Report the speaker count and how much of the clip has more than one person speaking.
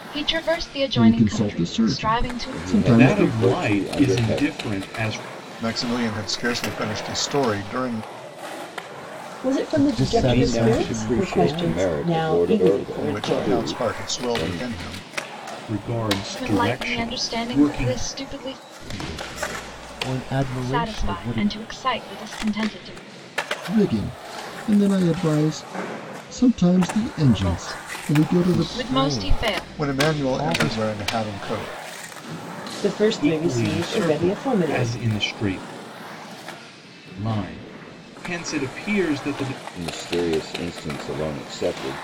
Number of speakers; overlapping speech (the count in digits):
7, about 39%